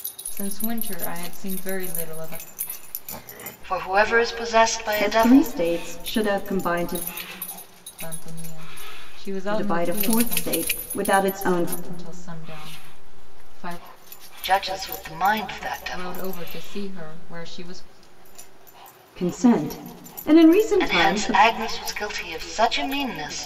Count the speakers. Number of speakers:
3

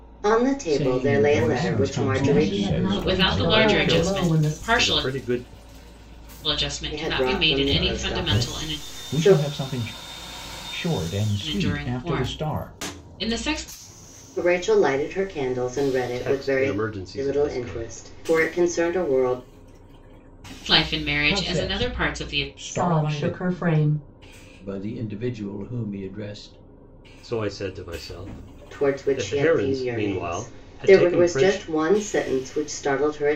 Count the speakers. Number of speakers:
6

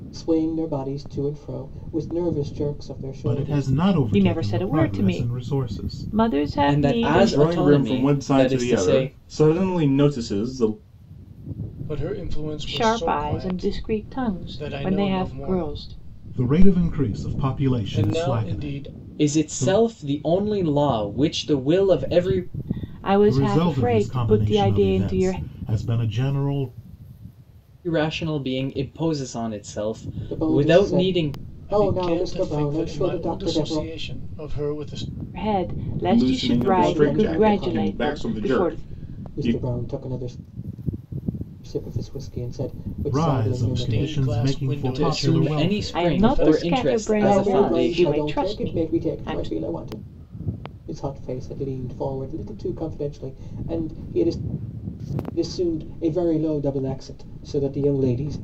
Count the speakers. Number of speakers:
6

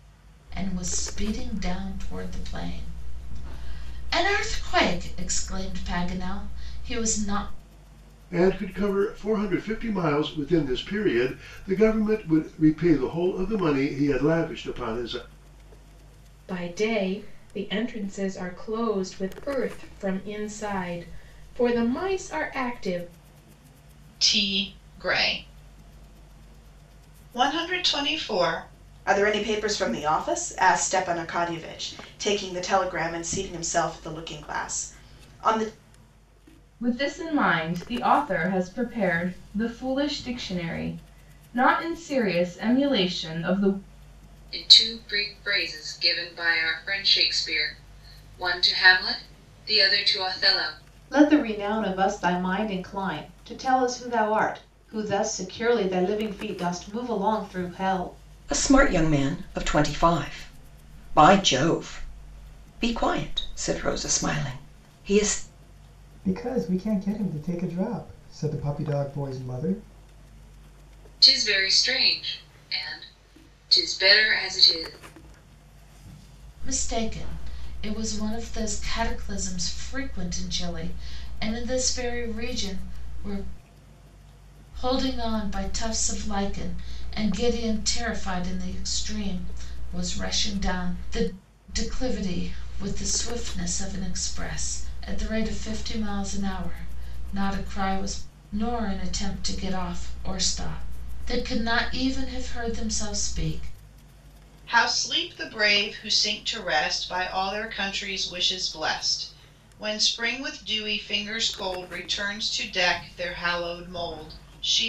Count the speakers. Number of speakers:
10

